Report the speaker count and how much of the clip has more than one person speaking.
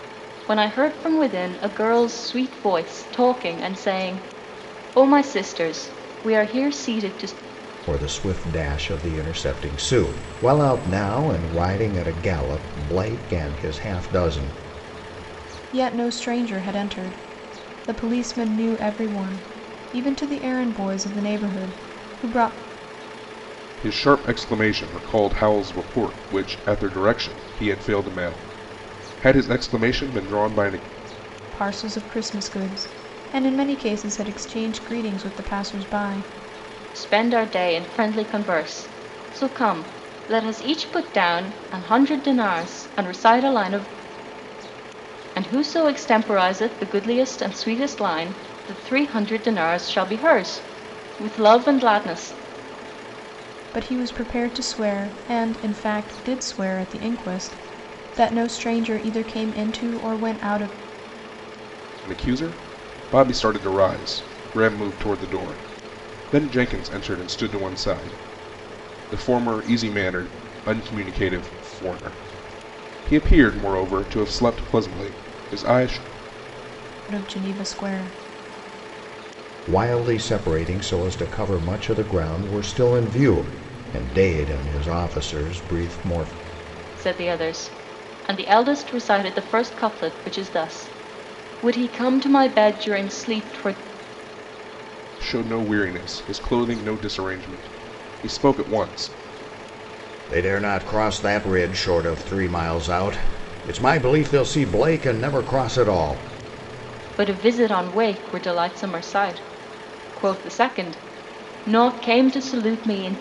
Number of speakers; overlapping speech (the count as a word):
four, no overlap